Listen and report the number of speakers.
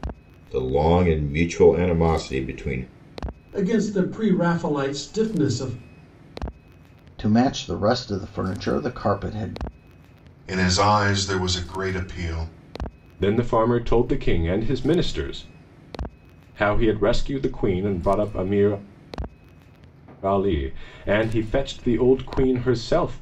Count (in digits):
5